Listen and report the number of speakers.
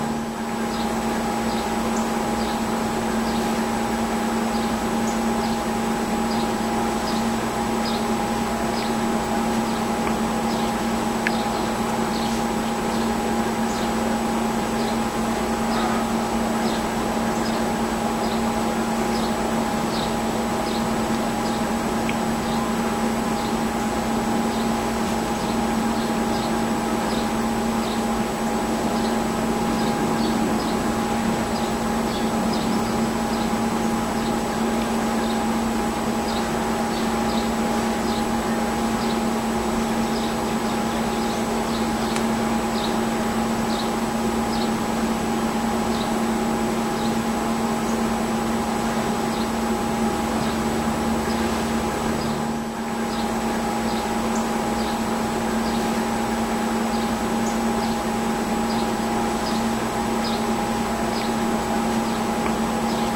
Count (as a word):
zero